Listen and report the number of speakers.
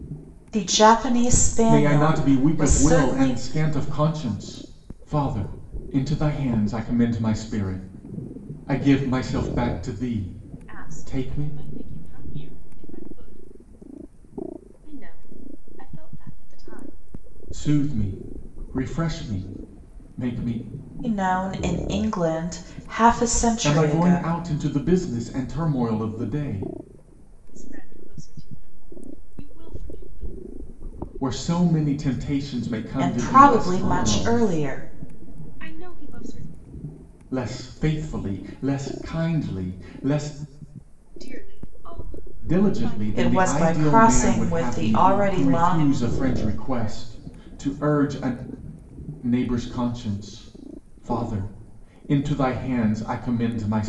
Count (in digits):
3